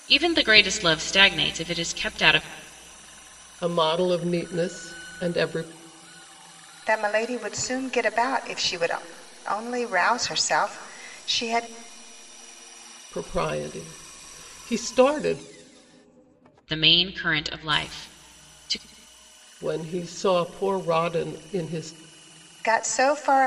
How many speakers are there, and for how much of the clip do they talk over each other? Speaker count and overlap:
3, no overlap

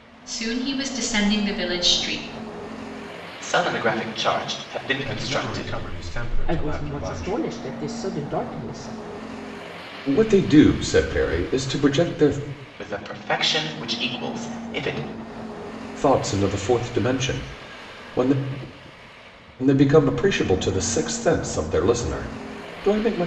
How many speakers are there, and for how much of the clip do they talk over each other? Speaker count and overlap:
5, about 7%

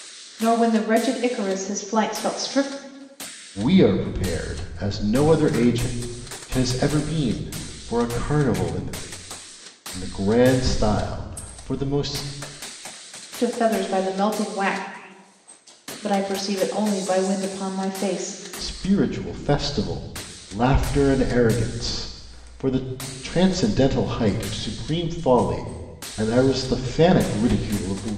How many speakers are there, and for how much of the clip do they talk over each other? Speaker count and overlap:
2, no overlap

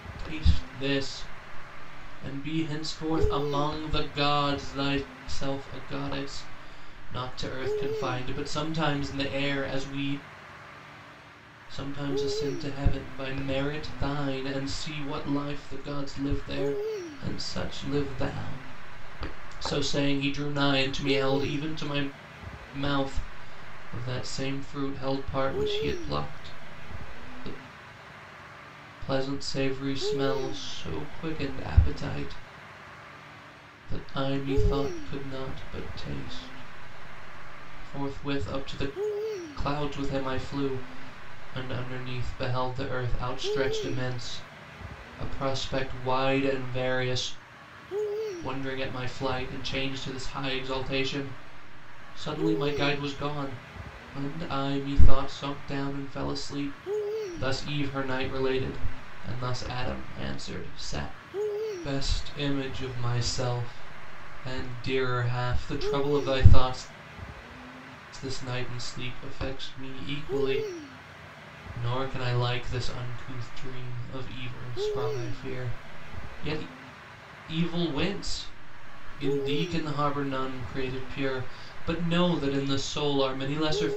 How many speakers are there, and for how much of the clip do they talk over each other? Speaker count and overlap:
1, no overlap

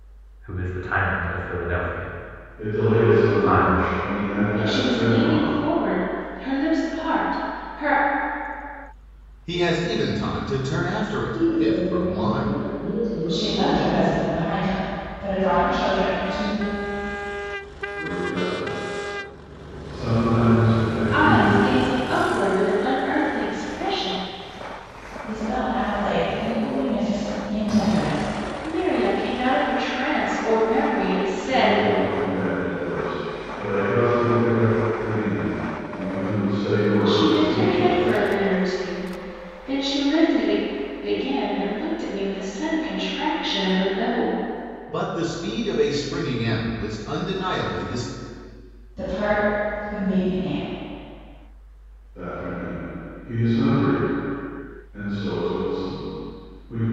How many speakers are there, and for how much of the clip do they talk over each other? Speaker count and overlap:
6, about 12%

